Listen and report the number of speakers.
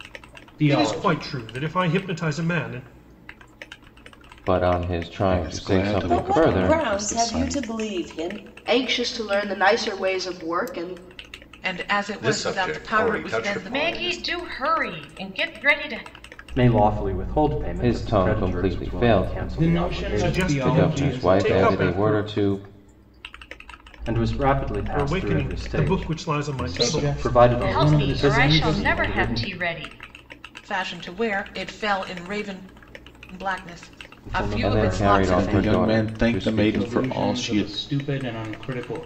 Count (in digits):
10